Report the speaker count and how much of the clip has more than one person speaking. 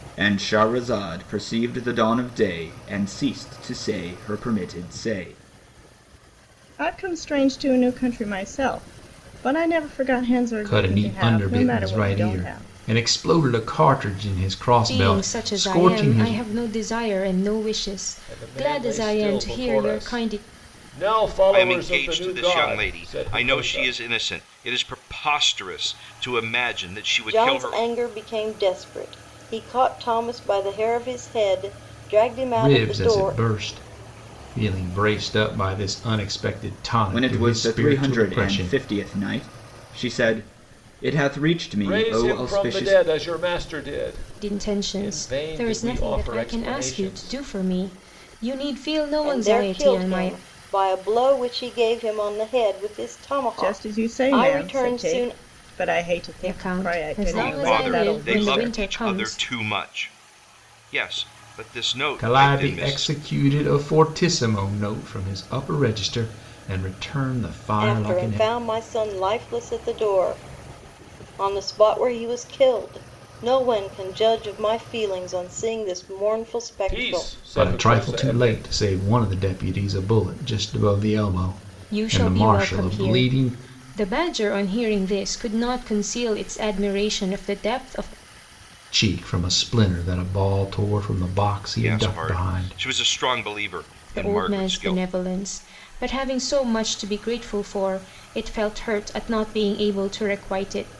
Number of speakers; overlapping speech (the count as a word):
seven, about 29%